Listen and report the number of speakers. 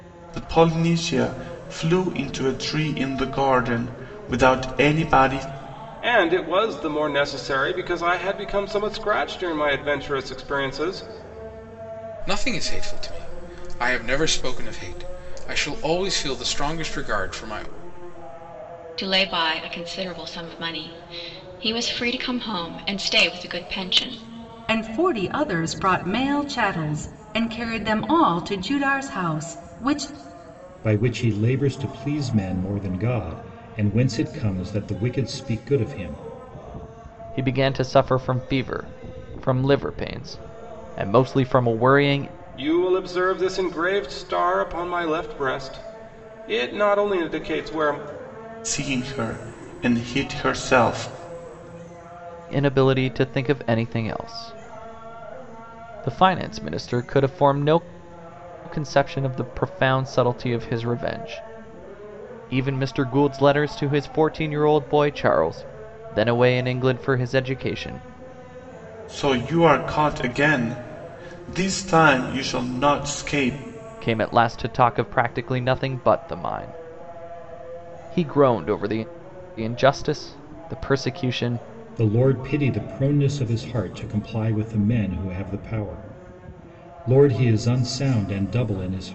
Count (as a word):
seven